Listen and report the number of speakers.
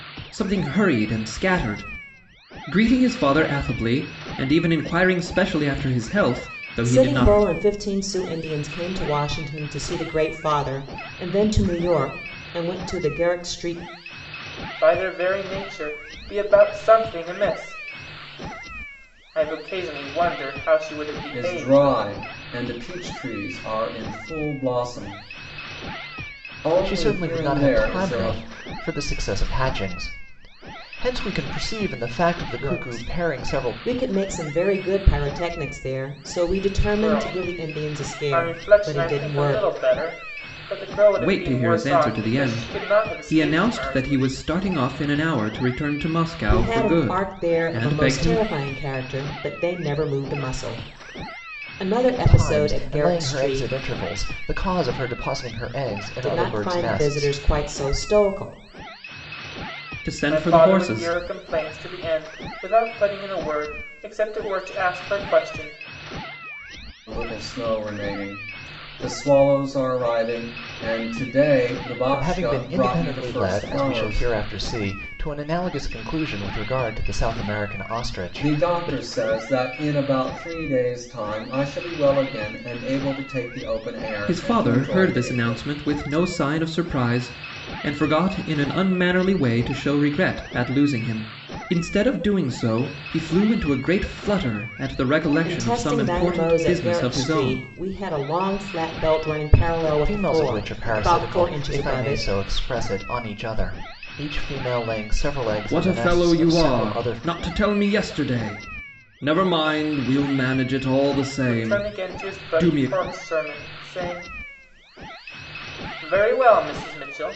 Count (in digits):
5